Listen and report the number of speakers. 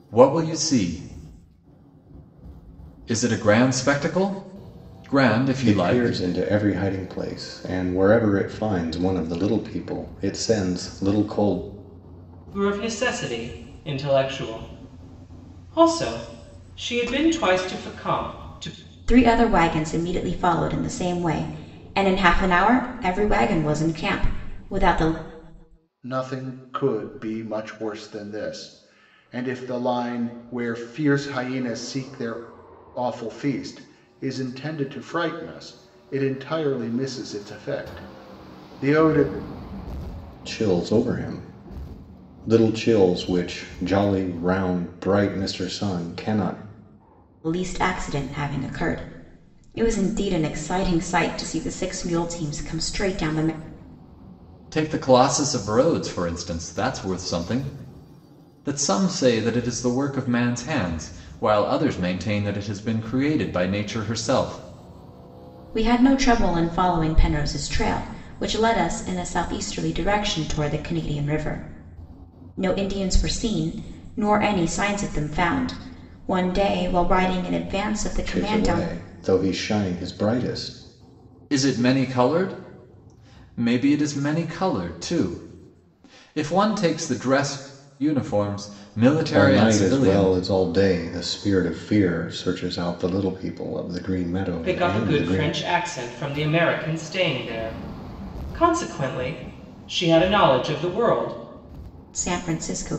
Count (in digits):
5